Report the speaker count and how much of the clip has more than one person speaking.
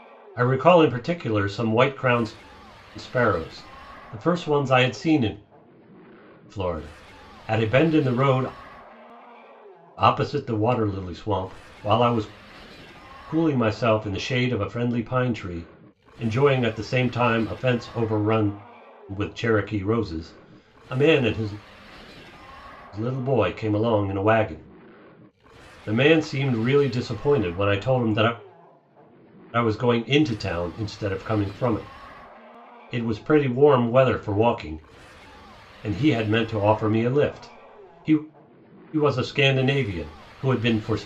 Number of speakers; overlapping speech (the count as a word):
one, no overlap